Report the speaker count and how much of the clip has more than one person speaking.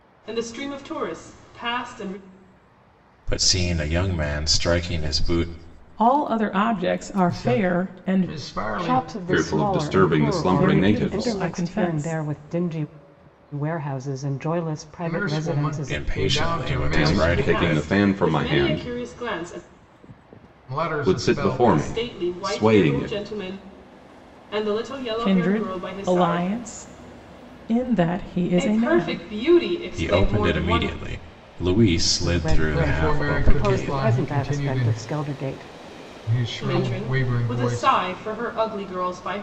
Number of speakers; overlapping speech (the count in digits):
6, about 46%